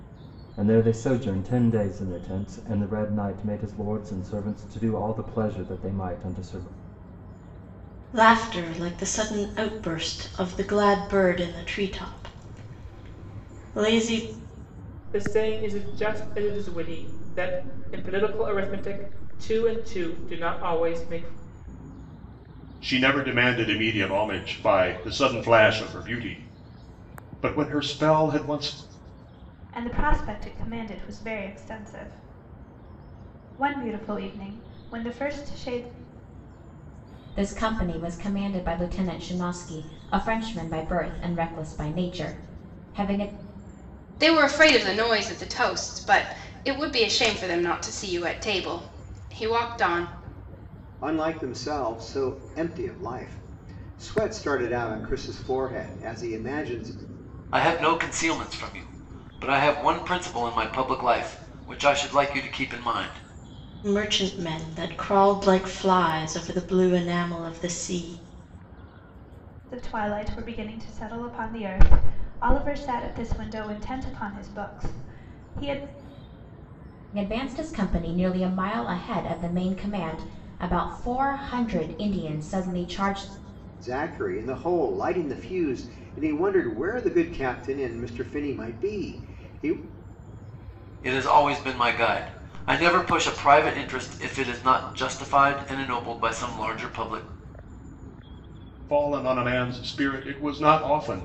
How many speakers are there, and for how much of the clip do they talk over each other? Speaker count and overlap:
nine, no overlap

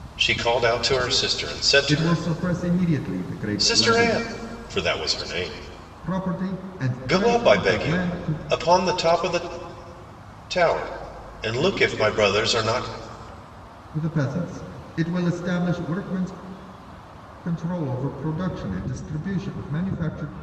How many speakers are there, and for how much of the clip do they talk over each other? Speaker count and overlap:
two, about 12%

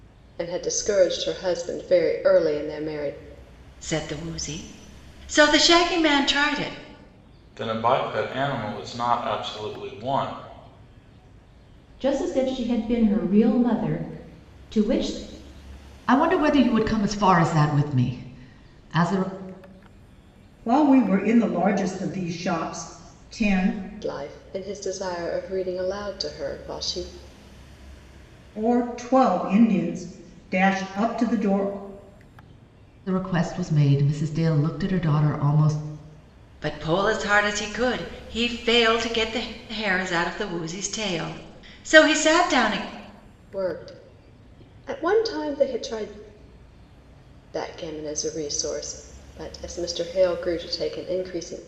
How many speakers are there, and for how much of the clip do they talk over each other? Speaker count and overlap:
six, no overlap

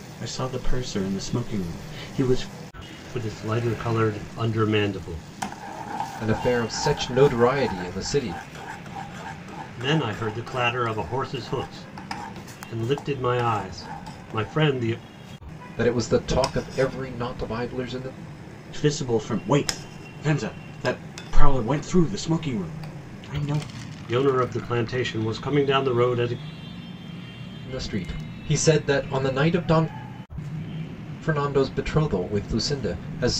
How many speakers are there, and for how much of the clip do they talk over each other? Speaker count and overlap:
three, no overlap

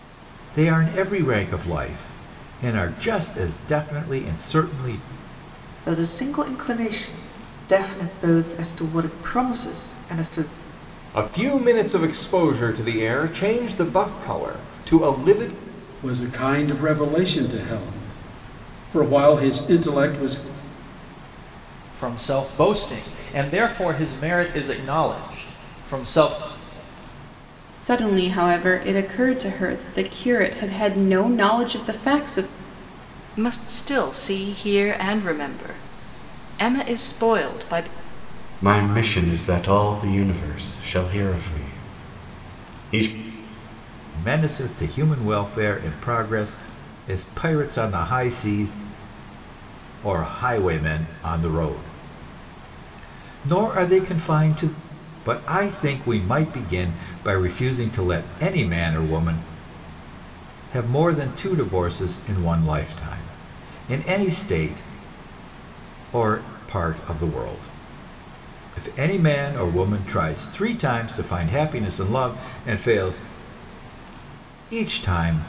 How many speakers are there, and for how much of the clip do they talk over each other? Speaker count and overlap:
eight, no overlap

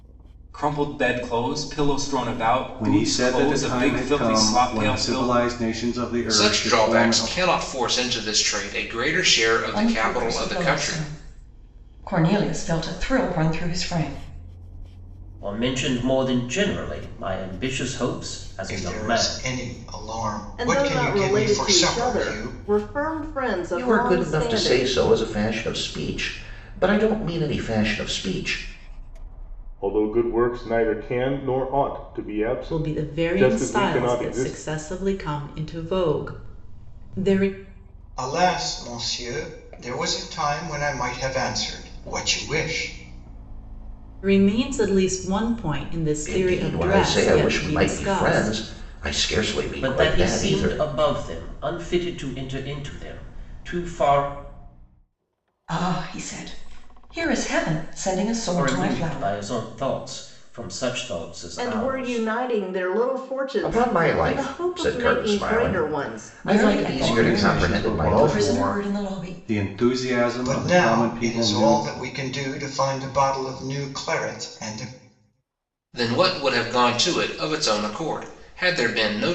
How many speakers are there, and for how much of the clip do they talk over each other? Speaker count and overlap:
ten, about 29%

